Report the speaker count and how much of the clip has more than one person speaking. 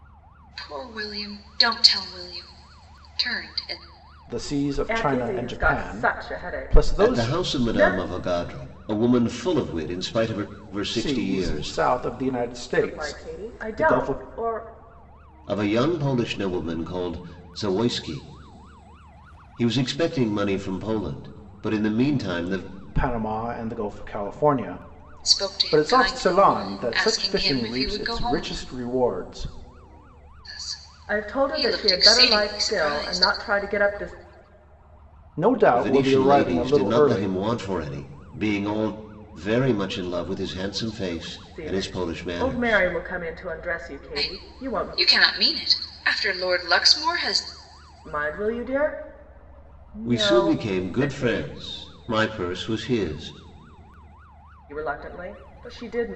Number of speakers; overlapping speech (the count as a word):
four, about 29%